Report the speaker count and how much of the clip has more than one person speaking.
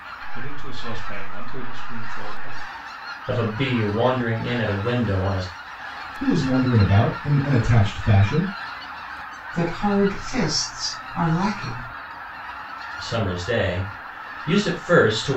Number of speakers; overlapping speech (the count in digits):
4, no overlap